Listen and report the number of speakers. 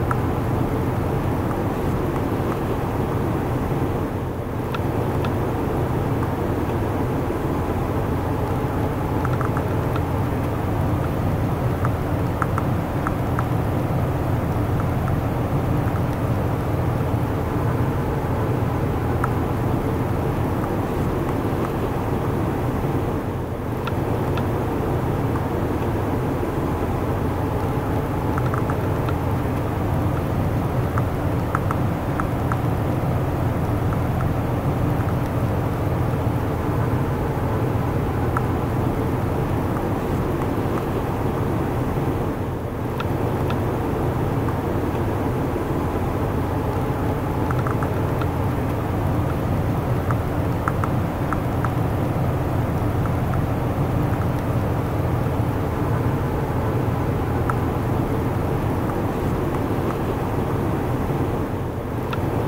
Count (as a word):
zero